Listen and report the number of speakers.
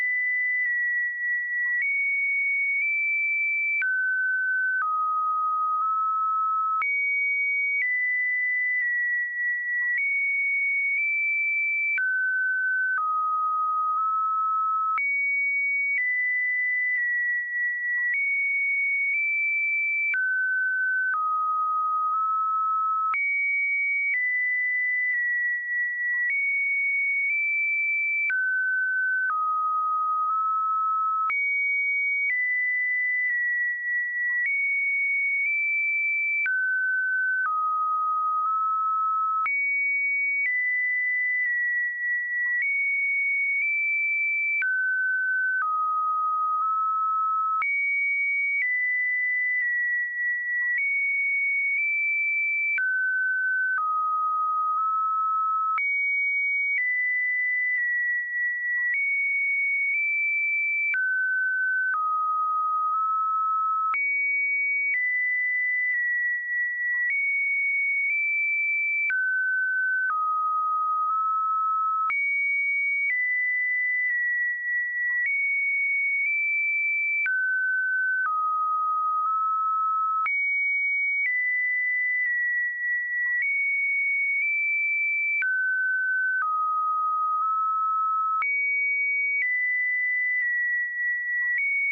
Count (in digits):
0